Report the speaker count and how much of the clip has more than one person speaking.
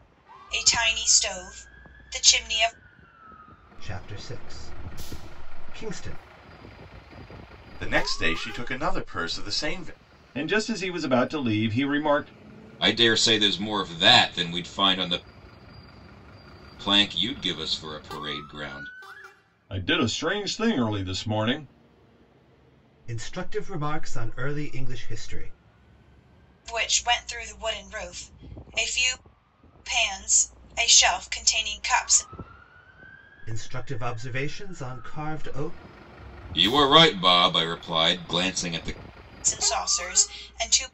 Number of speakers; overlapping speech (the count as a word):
five, no overlap